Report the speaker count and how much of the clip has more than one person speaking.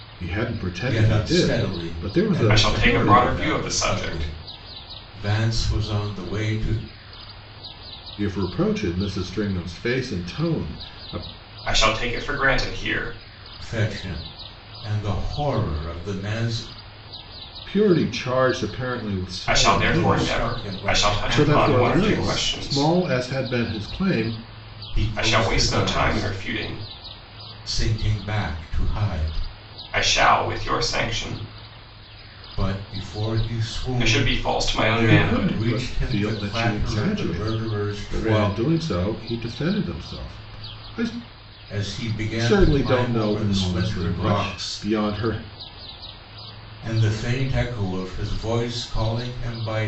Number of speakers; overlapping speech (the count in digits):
3, about 29%